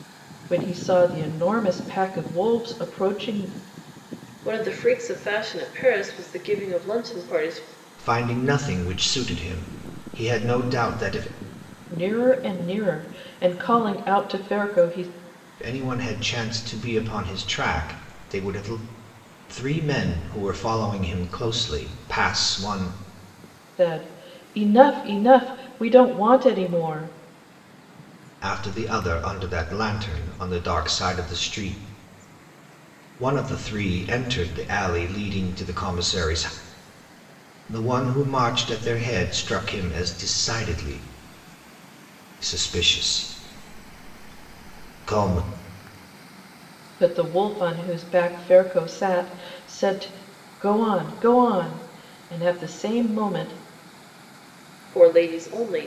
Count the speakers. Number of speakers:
three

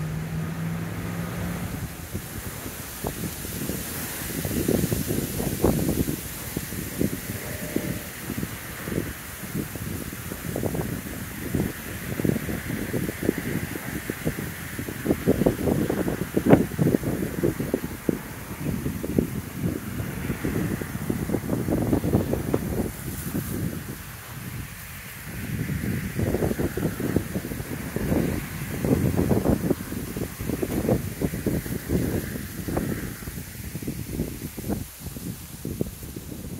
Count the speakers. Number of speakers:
zero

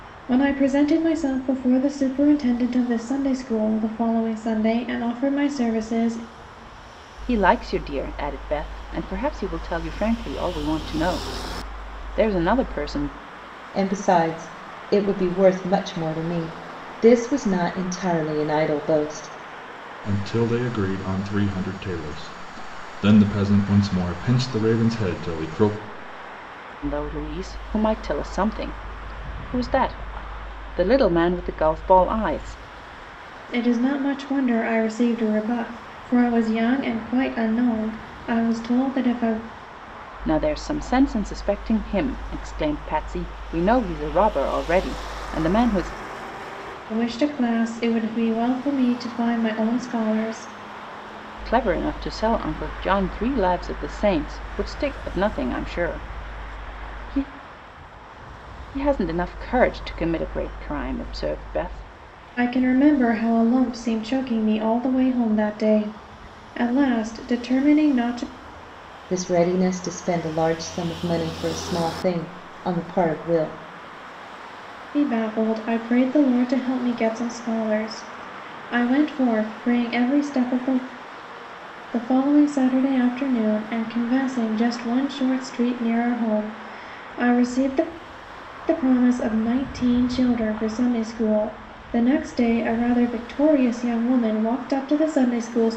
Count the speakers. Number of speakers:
four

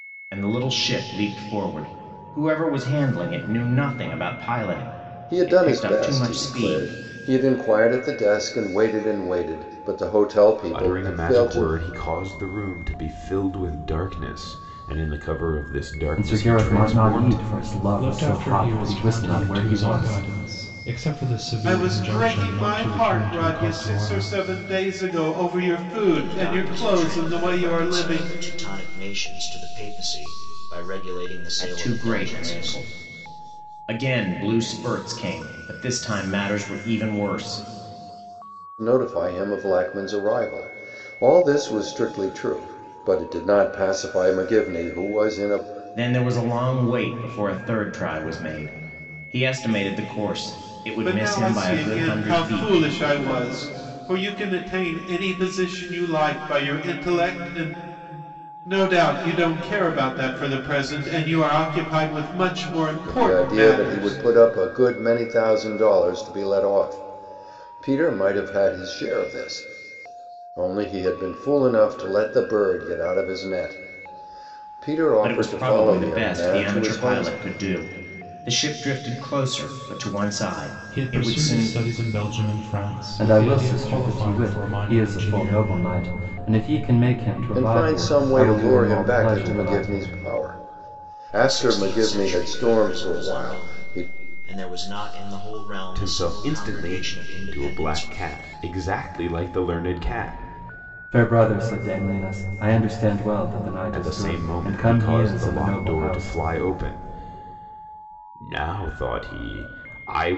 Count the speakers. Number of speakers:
seven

